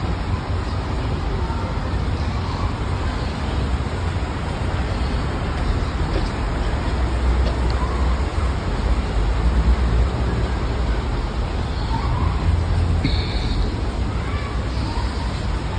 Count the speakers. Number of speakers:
0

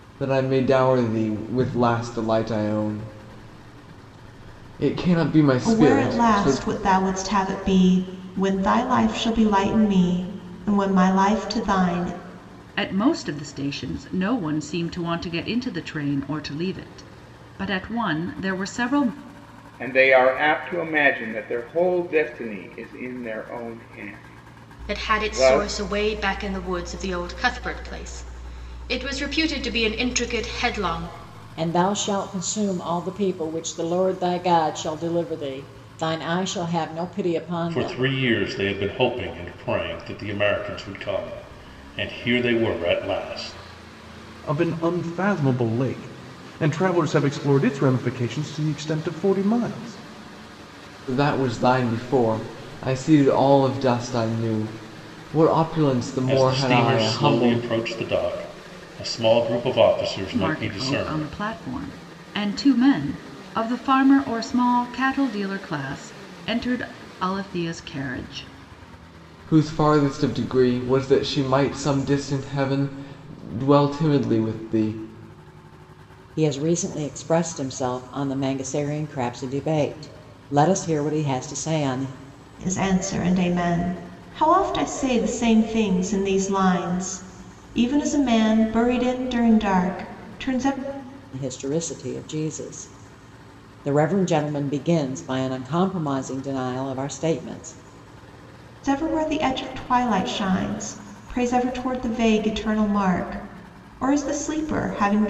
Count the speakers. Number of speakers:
8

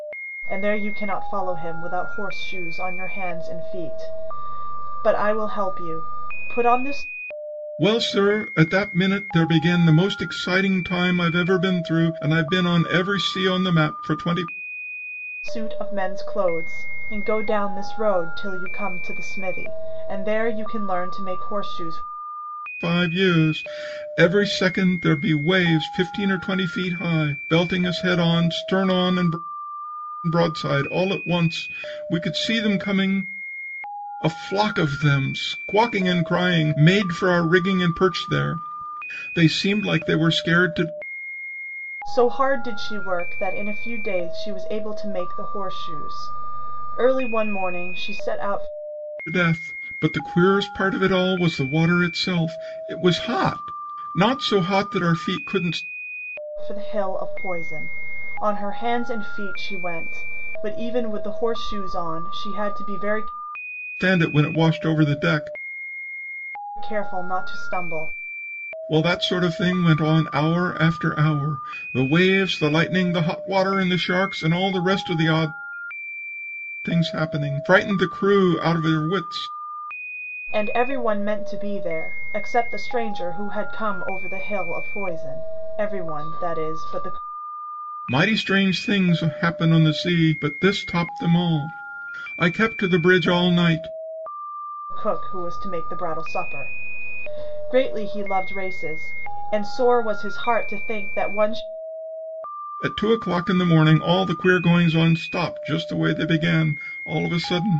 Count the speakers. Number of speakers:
2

